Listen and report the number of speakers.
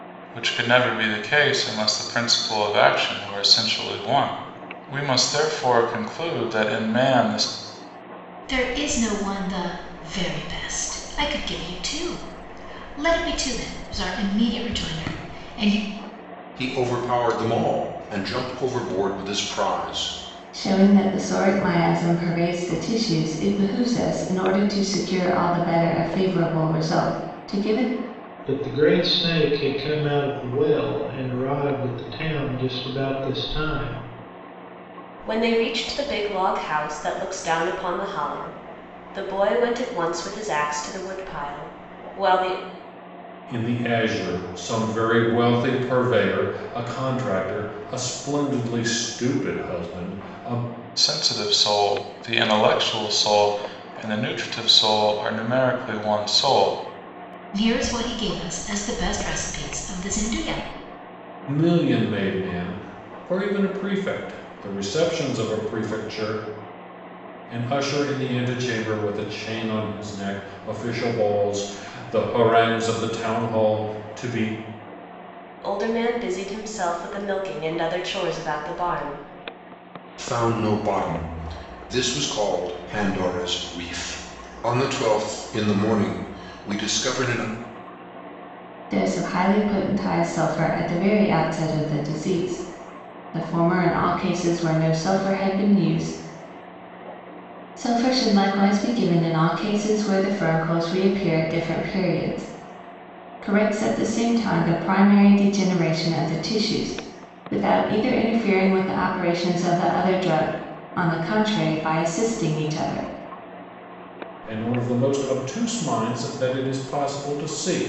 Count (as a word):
seven